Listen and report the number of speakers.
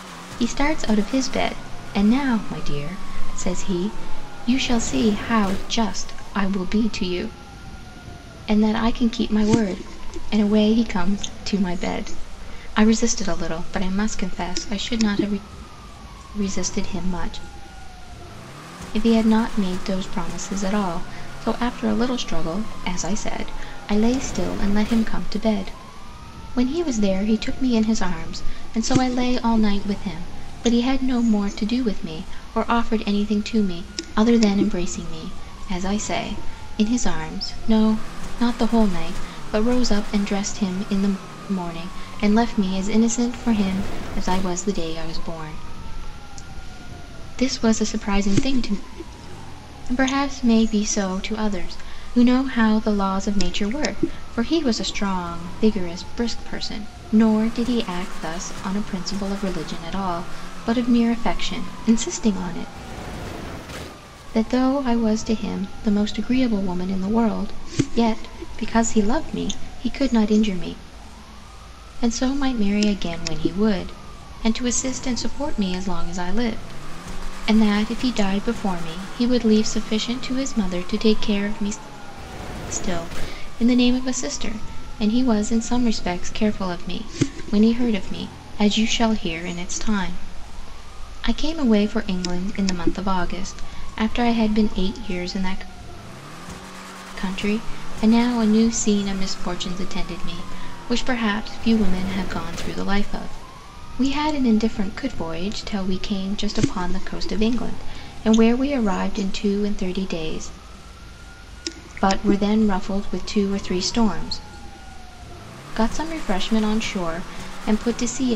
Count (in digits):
1